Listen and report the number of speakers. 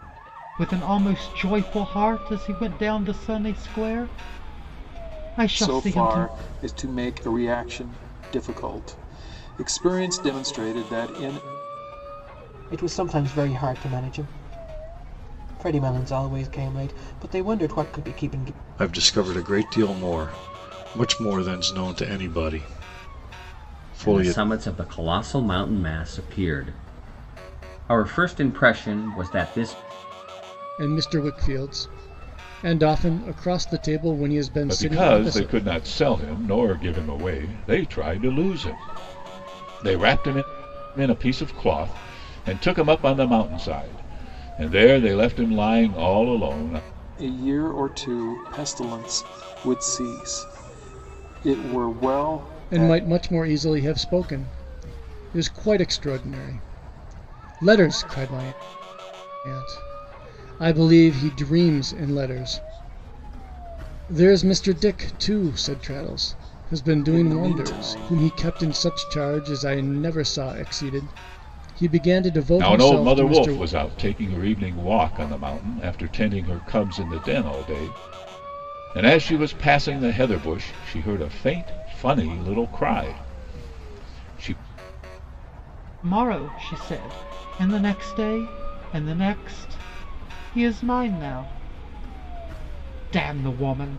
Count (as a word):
seven